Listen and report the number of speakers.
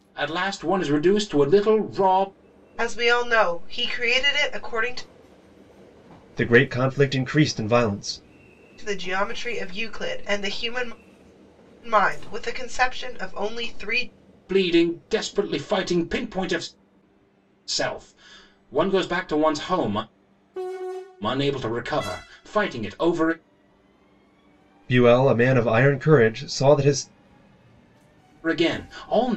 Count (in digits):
3